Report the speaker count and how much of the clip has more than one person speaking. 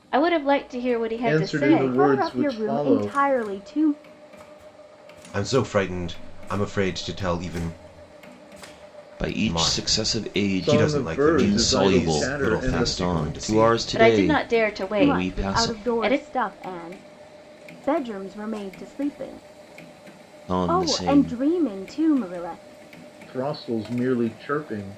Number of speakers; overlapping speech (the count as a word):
five, about 37%